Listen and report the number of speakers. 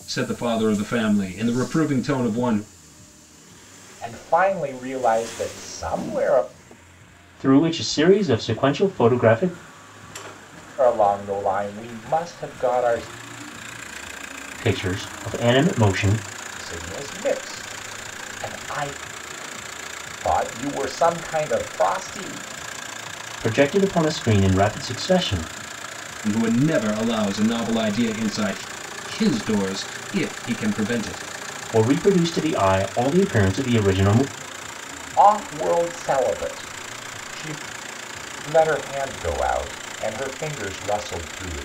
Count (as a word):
three